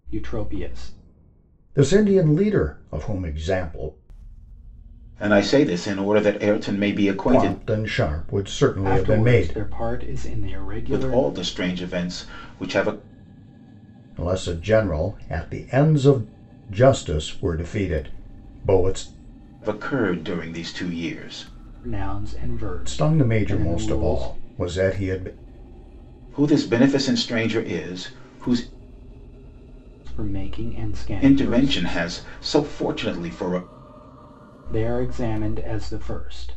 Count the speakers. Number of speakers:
3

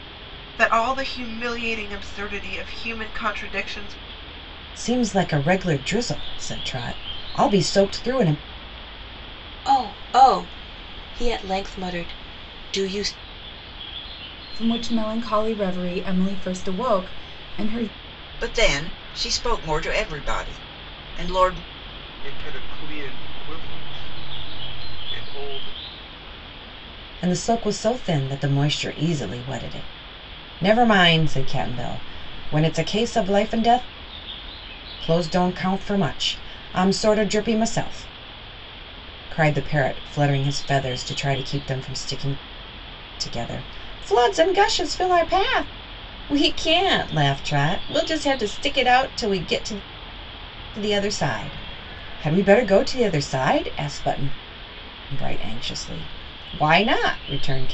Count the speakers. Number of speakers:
6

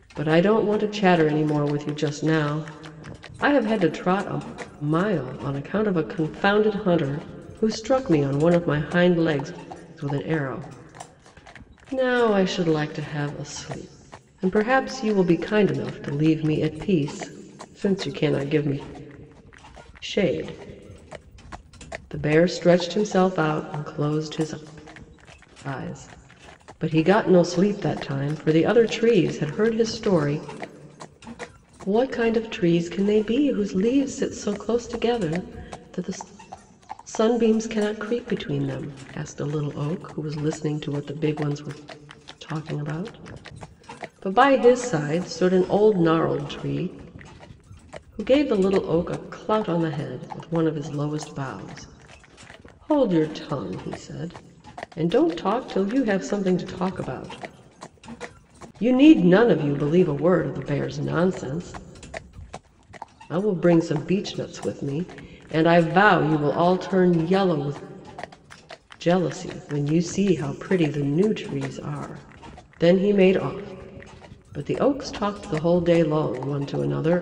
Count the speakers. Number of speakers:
1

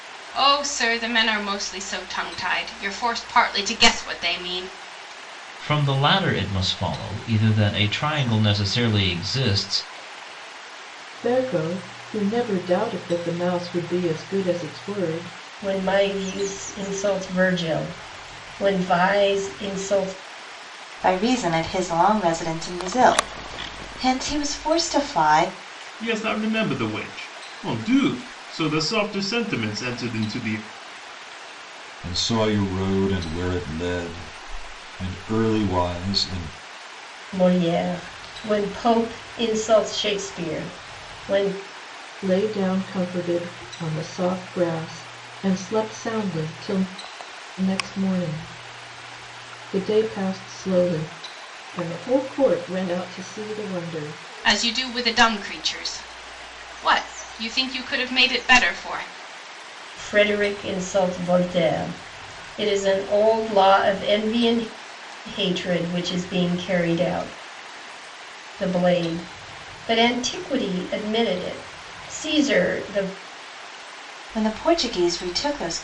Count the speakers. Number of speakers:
7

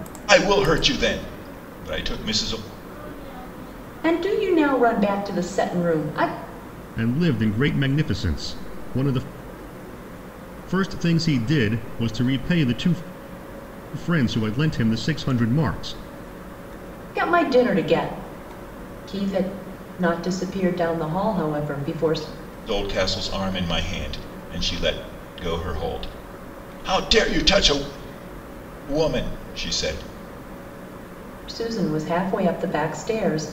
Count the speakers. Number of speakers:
3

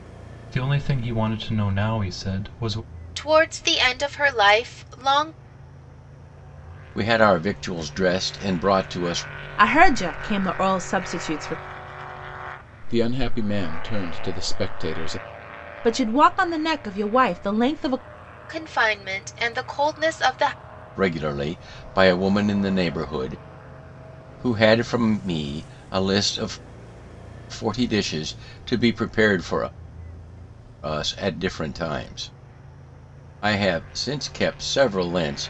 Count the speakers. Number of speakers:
5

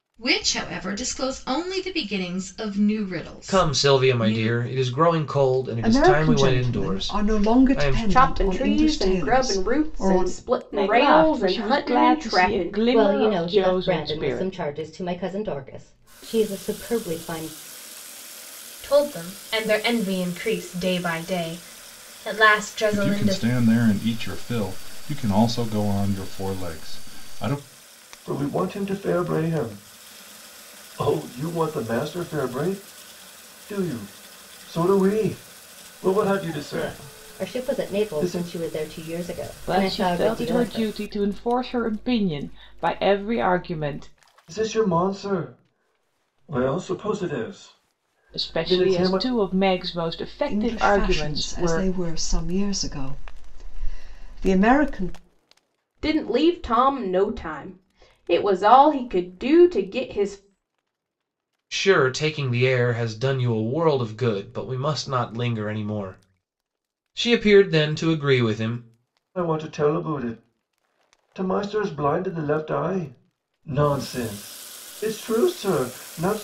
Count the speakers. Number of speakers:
9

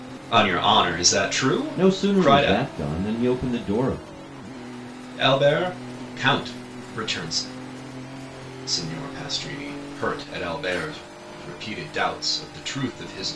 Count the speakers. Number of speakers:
2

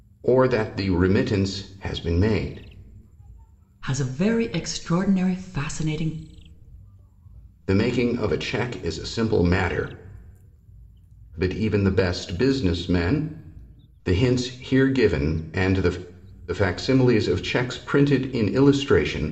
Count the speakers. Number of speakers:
2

